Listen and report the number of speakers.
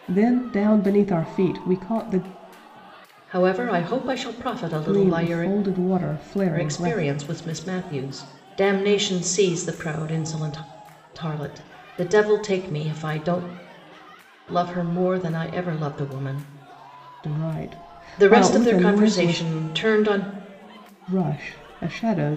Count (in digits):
2